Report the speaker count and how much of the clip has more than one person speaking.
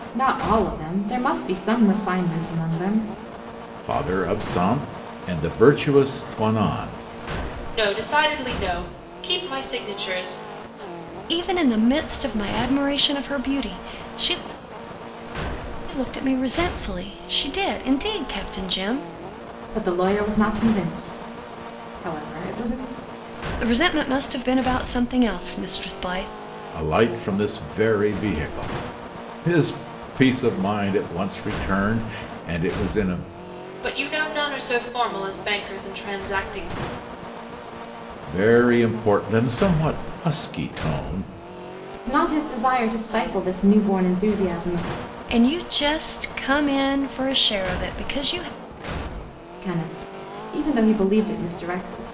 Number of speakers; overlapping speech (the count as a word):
four, no overlap